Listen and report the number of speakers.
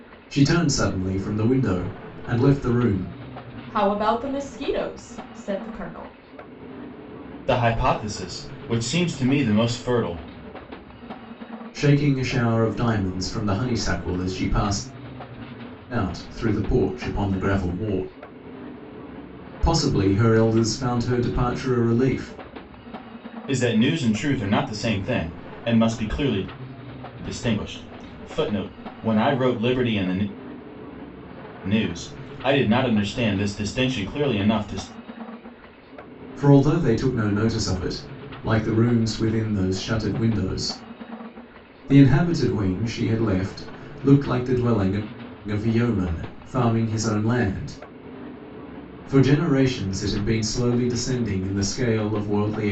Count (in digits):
3